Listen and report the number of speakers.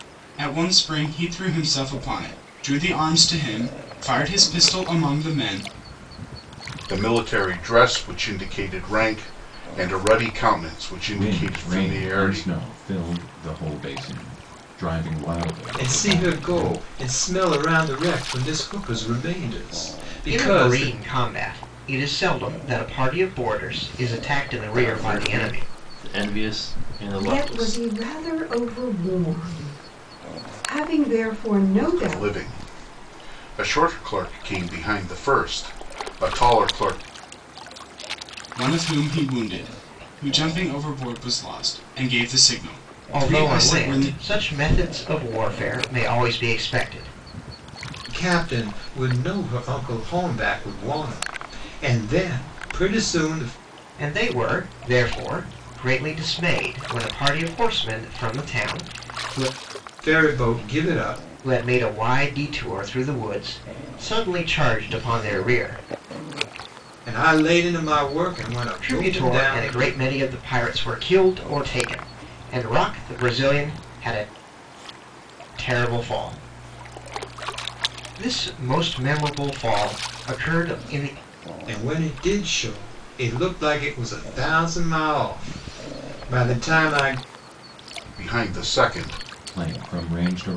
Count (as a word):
seven